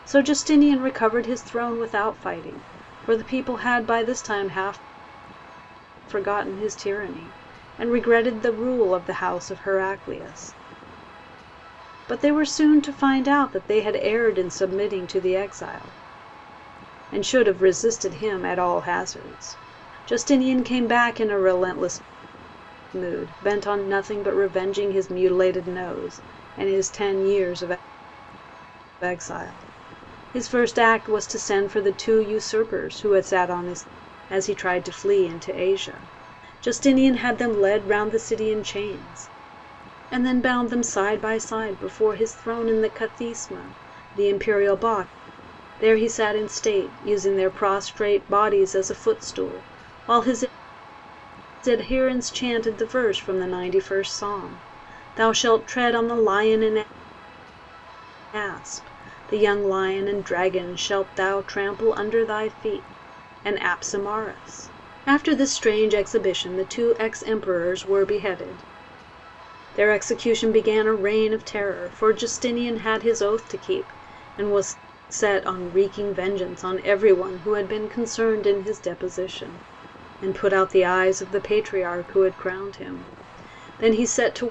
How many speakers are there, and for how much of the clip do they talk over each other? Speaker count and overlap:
one, no overlap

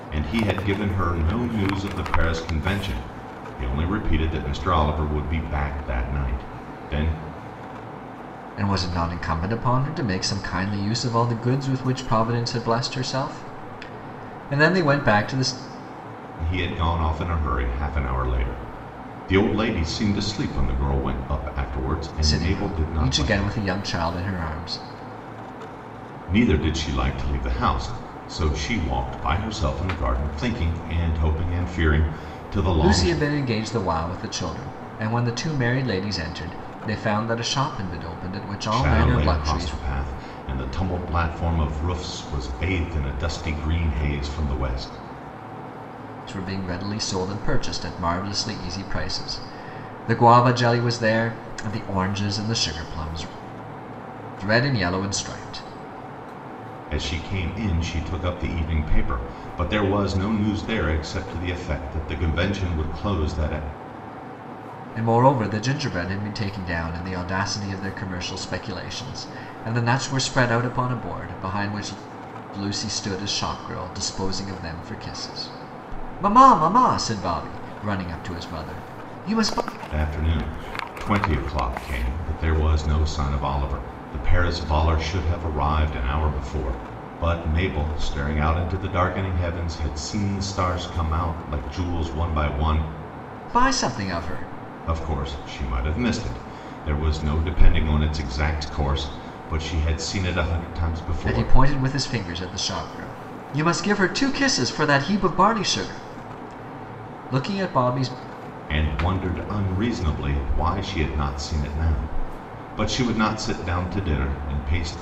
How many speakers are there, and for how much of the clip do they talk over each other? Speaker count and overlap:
two, about 3%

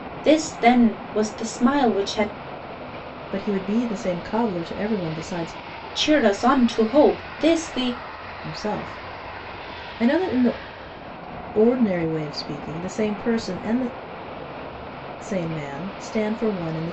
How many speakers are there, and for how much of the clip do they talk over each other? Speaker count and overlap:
two, no overlap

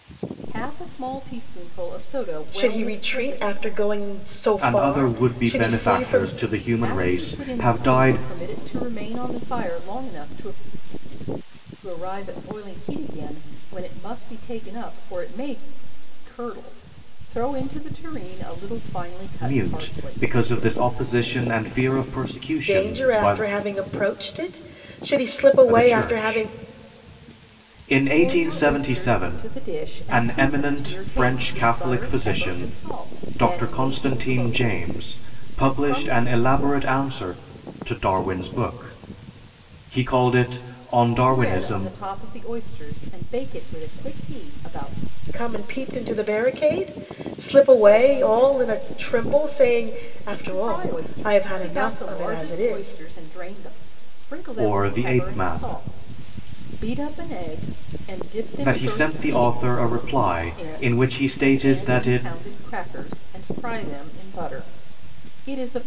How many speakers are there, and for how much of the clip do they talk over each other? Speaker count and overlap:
three, about 35%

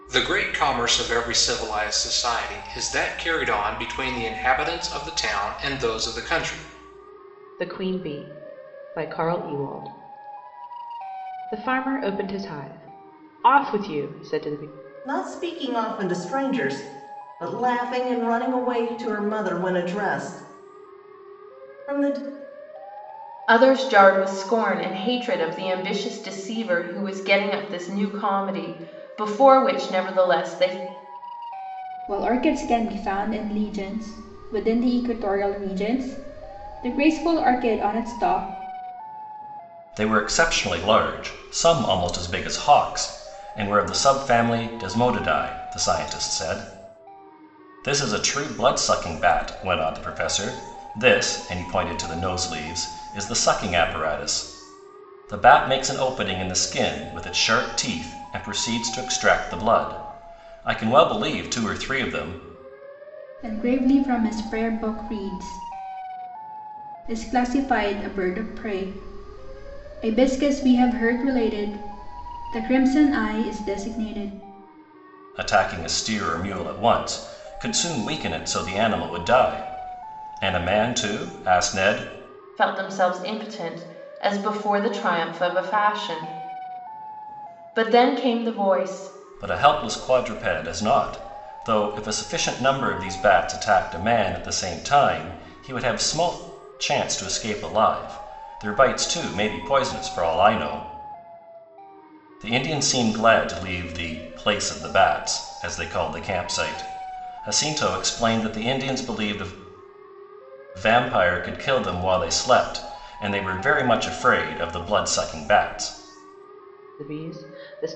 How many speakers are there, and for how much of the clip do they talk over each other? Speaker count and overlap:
six, no overlap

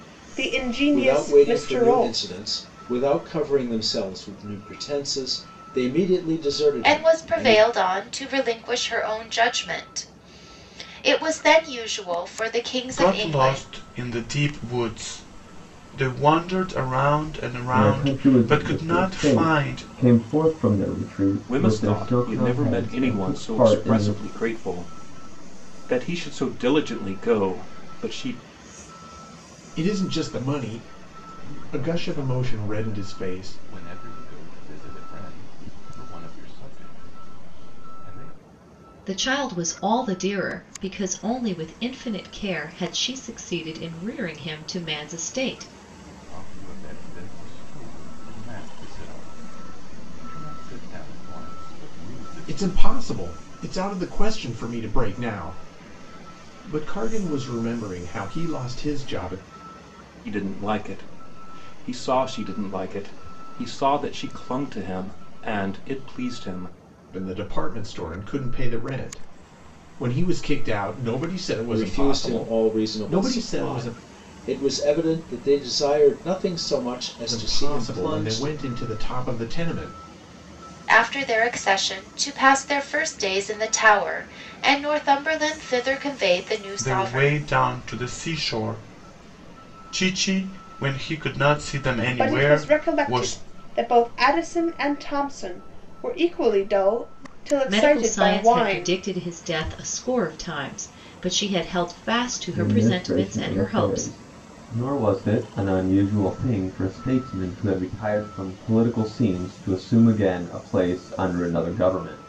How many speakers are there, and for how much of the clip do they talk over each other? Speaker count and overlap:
nine, about 17%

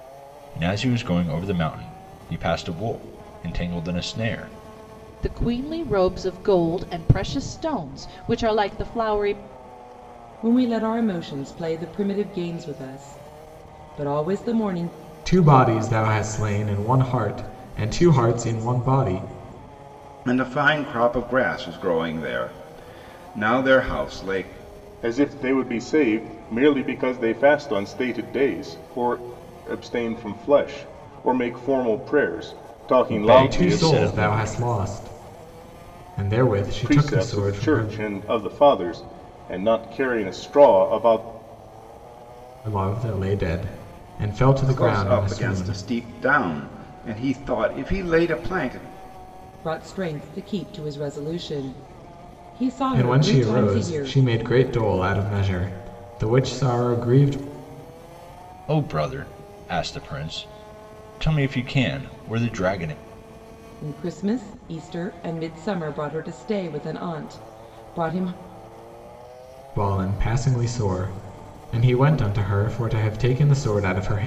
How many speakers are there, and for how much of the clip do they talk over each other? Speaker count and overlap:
six, about 7%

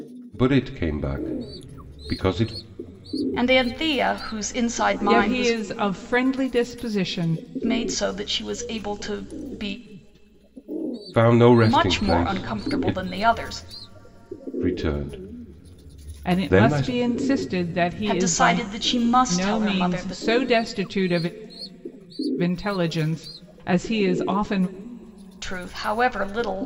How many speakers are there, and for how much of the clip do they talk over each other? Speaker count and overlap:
three, about 16%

